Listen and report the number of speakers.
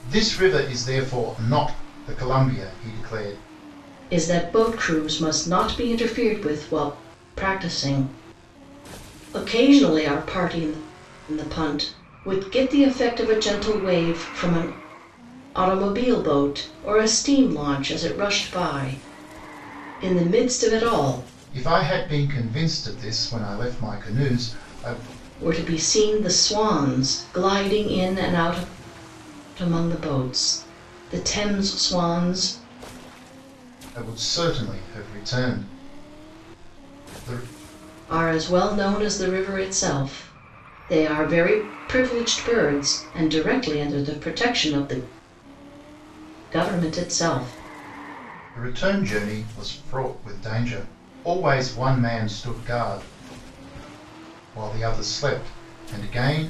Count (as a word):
two